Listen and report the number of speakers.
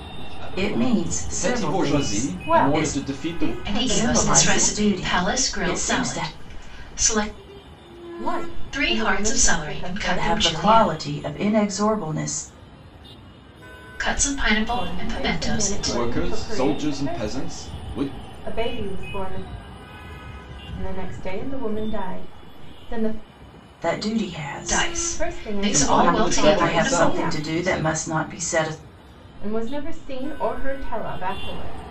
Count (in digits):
5